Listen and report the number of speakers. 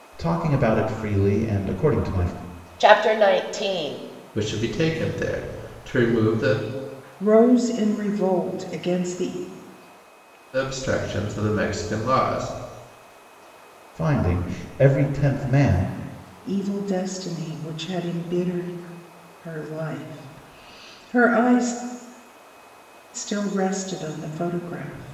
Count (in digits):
4